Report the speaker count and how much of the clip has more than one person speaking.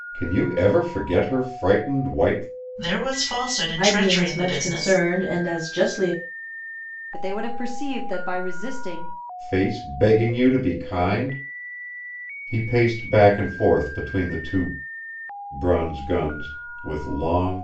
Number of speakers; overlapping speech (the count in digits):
4, about 7%